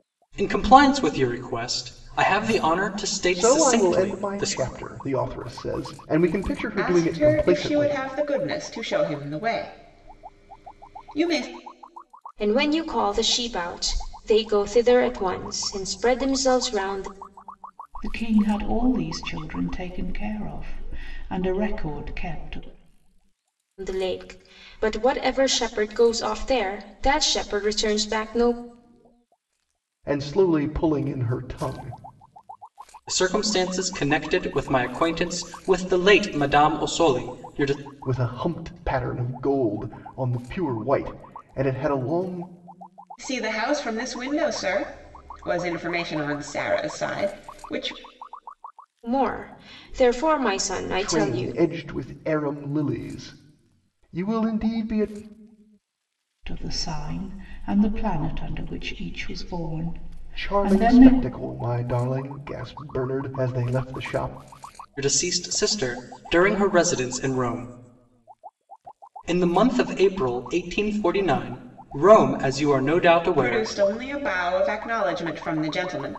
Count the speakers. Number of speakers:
five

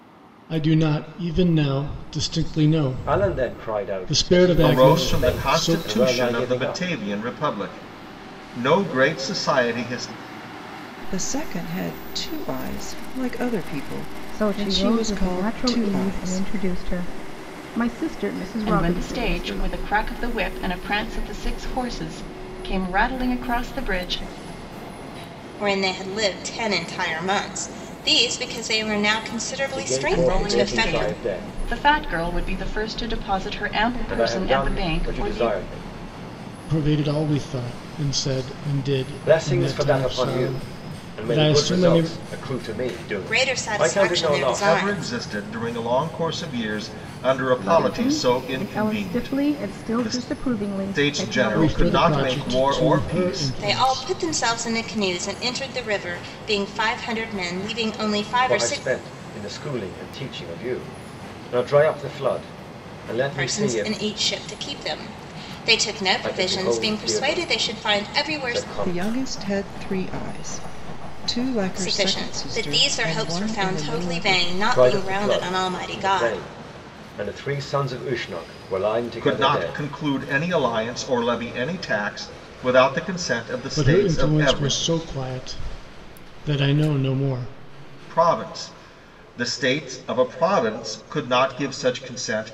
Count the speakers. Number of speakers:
seven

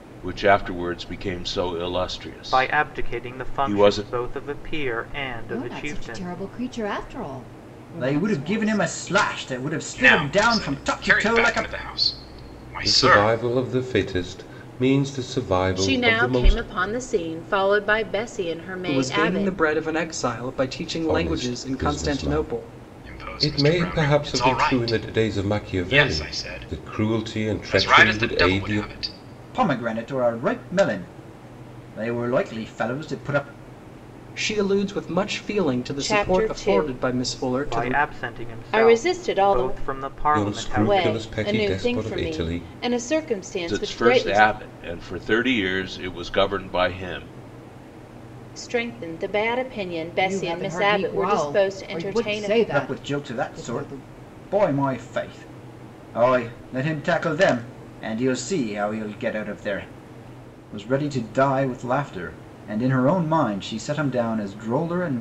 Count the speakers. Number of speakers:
eight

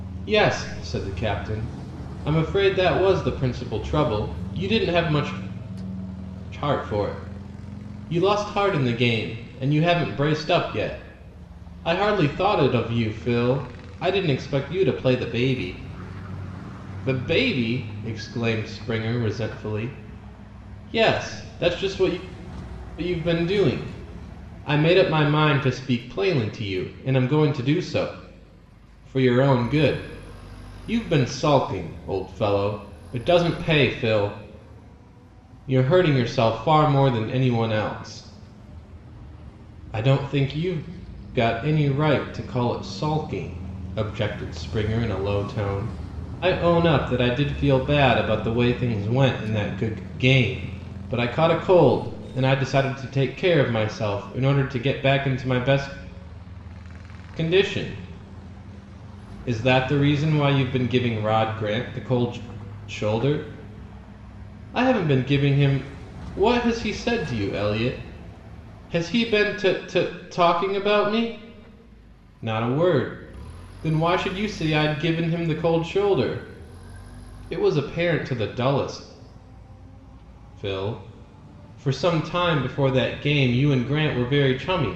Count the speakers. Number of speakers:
one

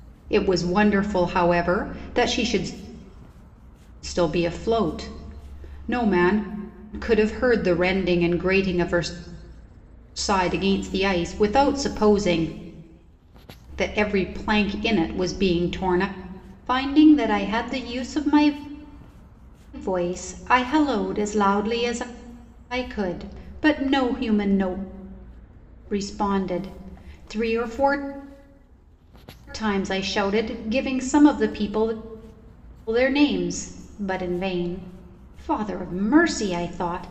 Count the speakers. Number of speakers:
one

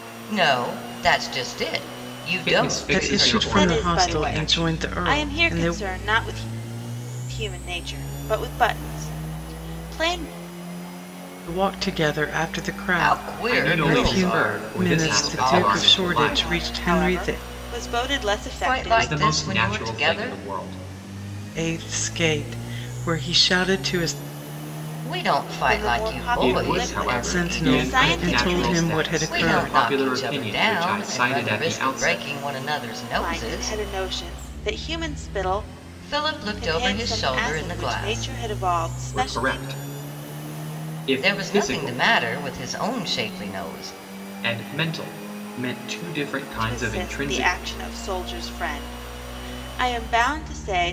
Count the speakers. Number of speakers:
four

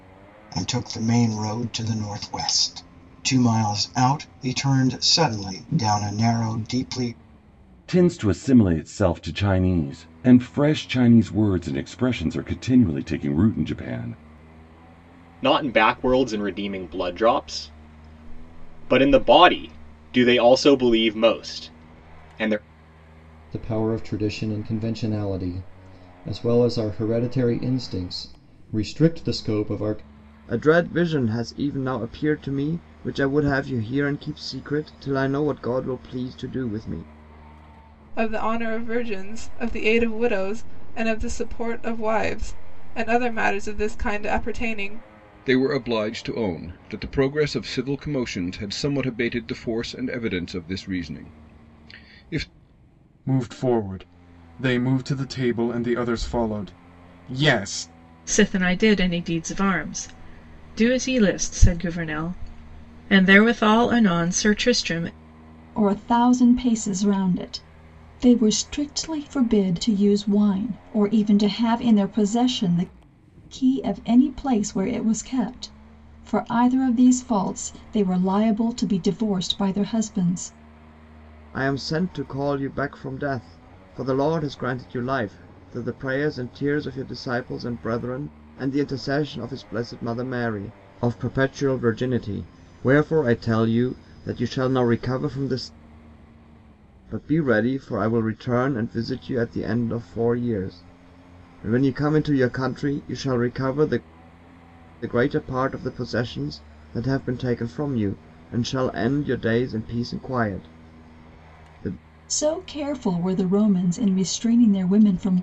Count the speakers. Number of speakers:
ten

